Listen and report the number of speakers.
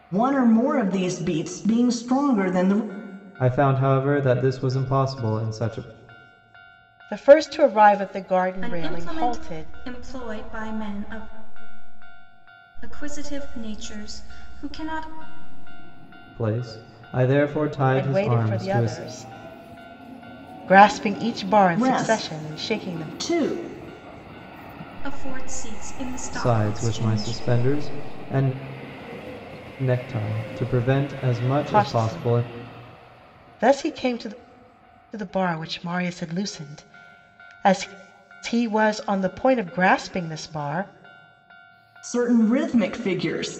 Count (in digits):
4